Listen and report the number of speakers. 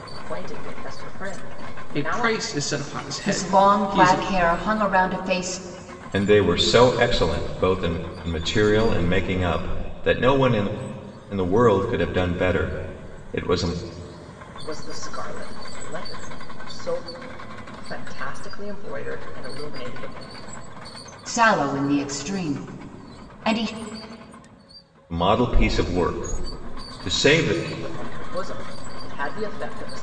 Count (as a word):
four